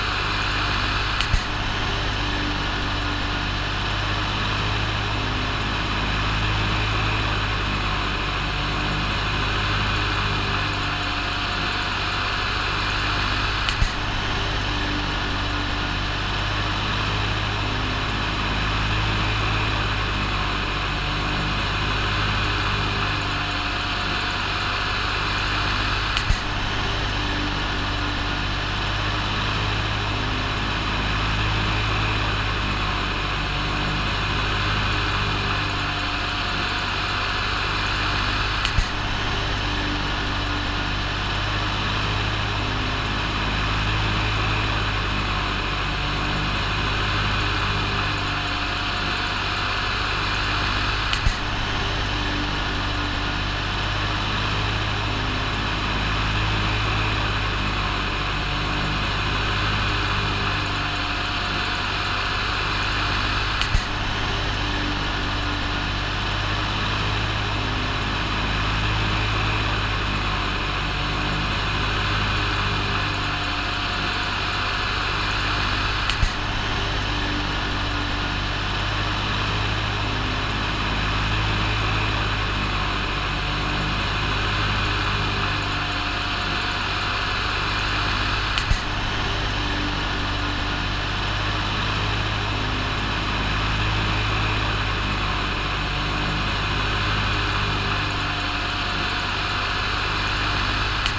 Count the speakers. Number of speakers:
zero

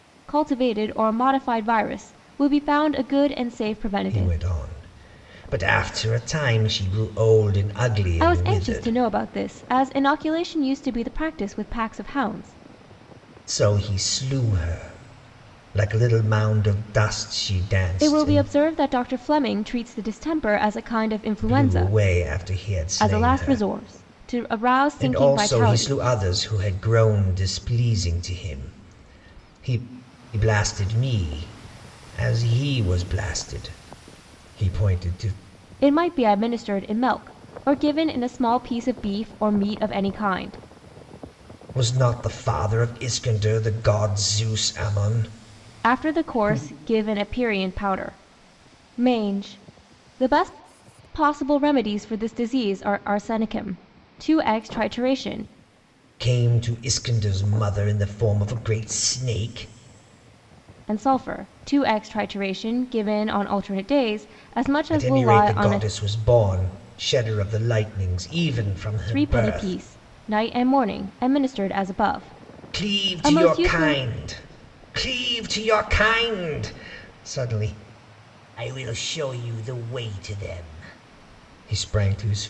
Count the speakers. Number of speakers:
two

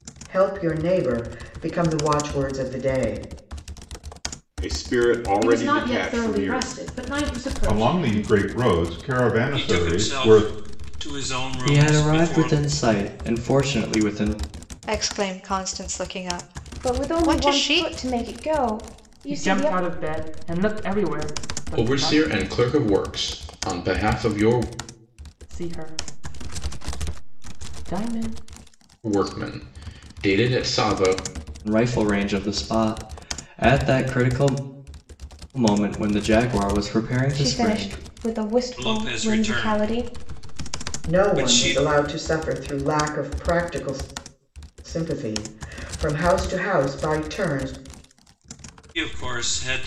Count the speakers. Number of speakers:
ten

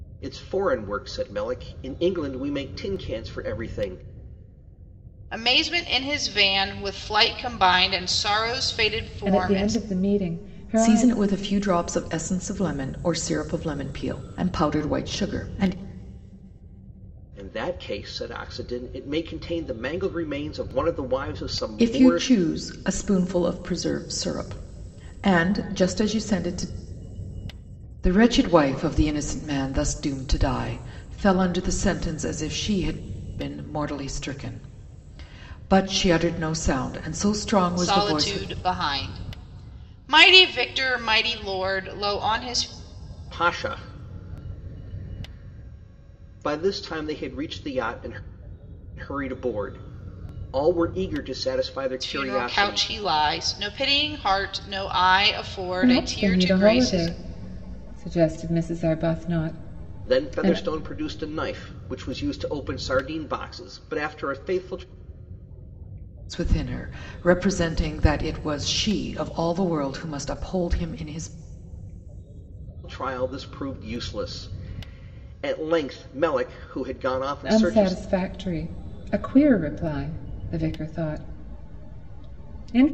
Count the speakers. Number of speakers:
four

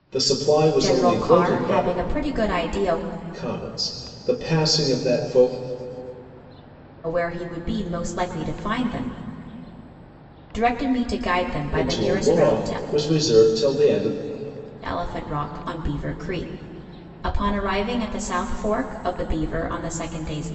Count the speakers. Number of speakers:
two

